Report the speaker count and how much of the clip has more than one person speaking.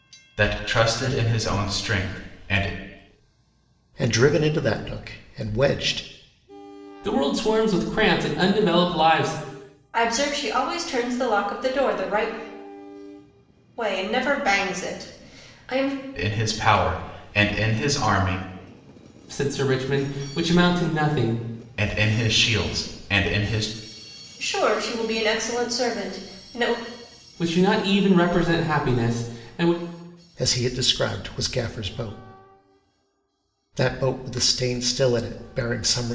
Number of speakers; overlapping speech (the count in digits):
4, no overlap